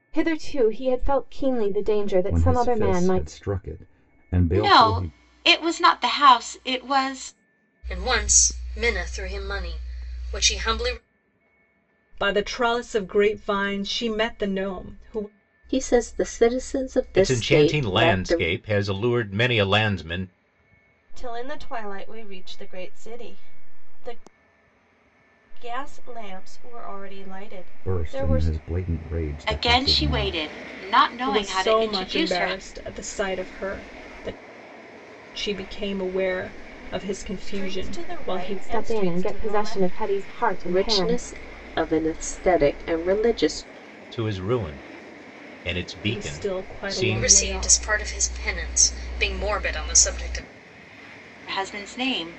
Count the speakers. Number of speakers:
eight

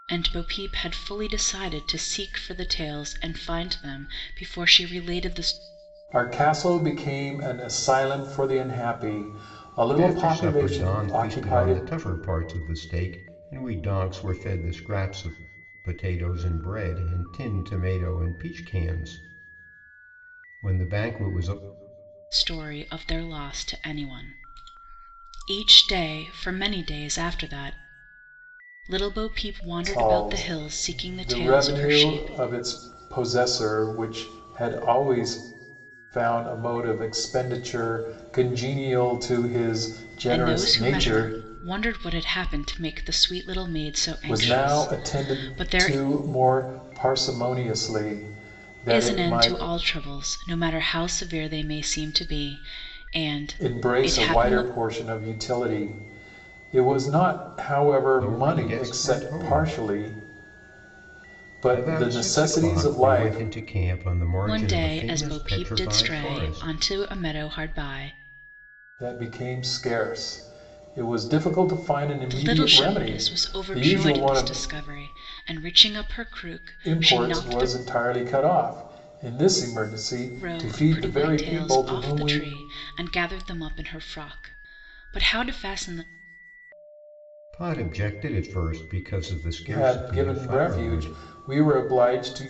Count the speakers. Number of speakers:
three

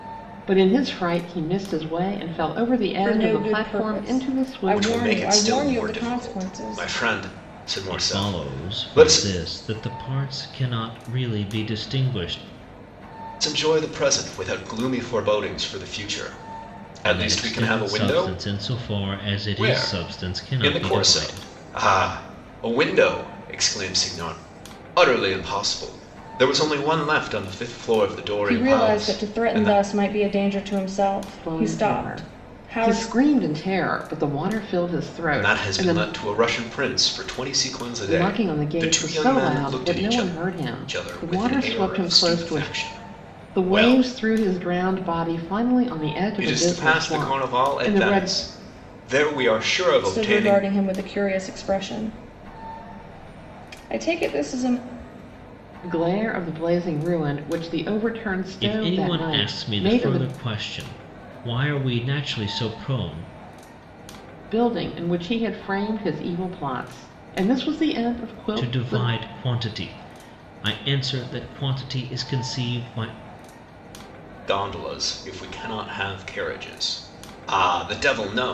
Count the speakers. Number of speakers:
four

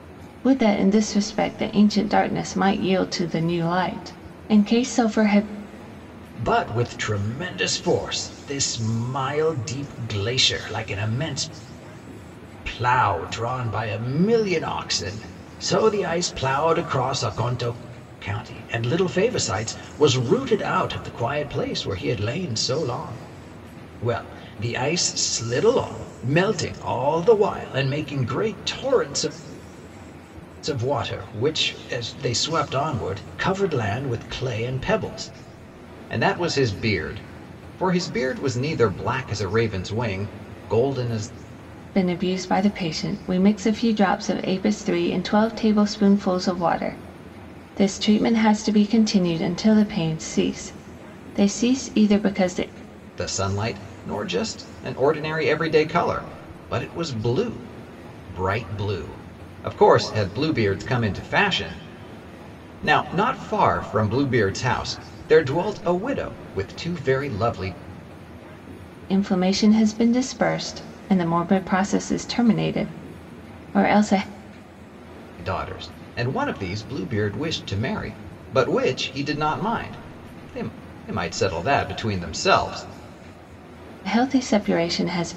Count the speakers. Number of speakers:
two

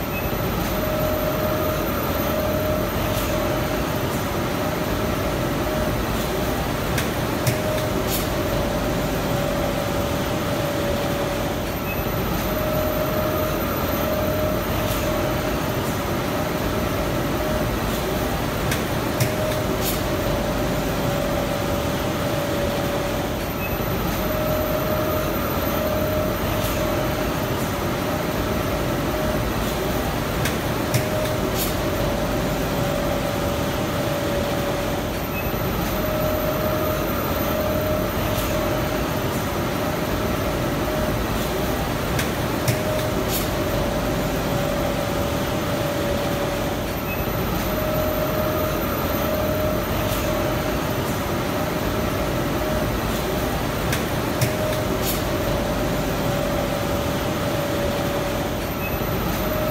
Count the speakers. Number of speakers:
zero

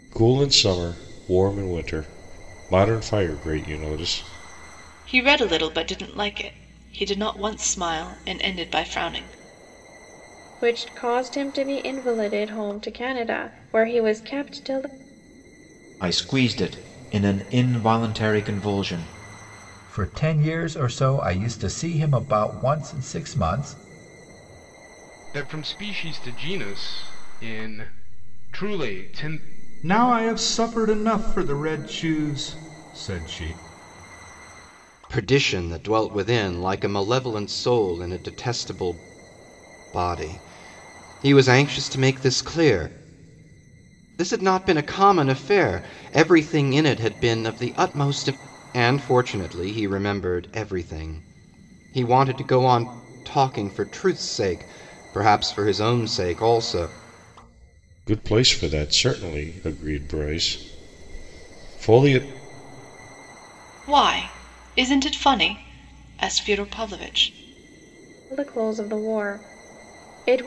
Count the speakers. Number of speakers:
eight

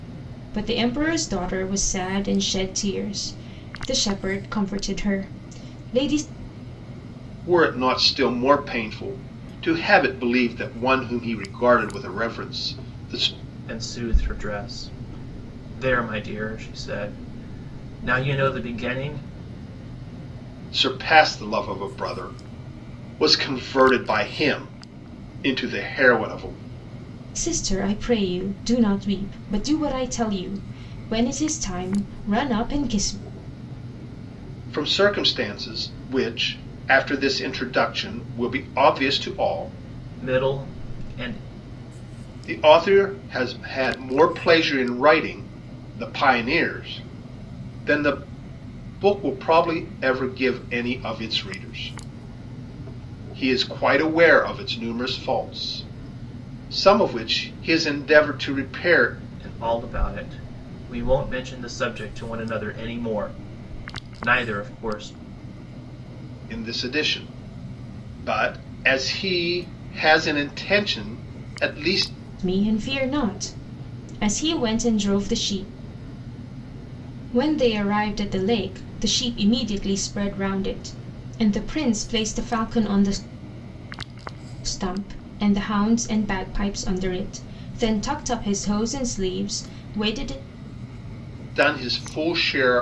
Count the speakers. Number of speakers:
three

